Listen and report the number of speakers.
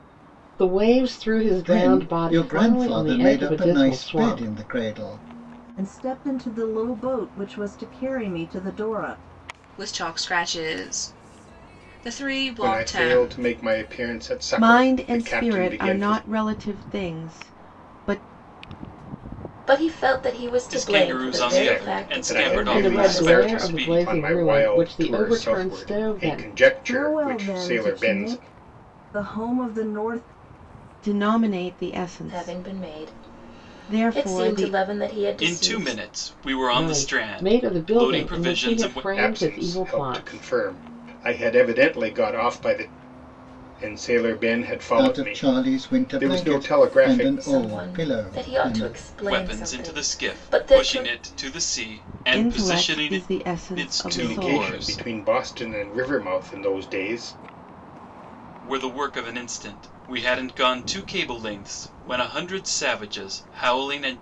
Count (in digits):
8